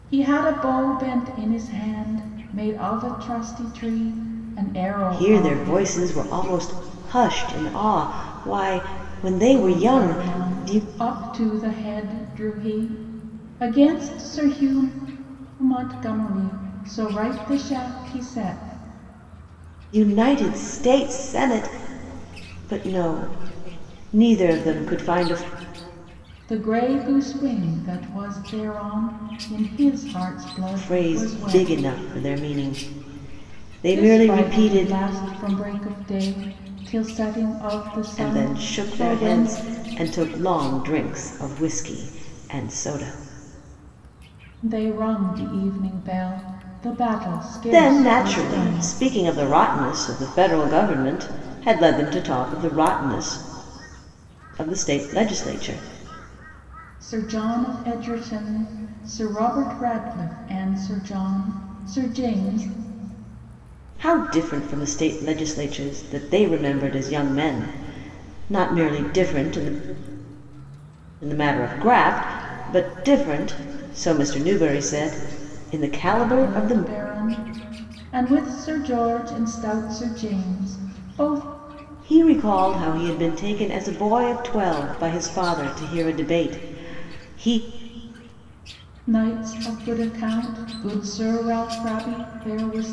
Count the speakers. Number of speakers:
2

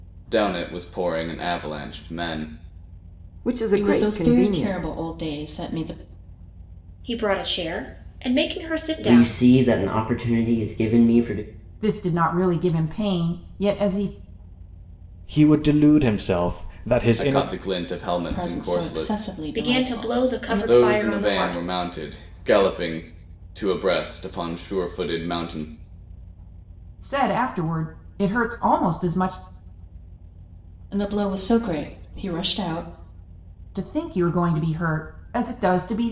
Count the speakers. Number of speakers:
7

